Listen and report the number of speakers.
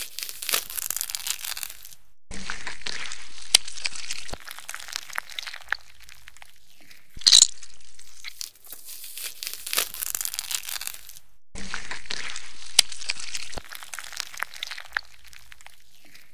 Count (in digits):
0